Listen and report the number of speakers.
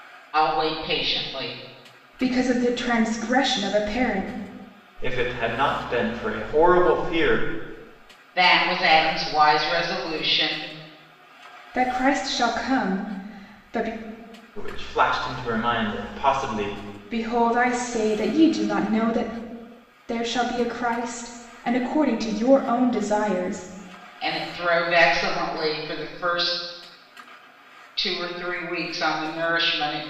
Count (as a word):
three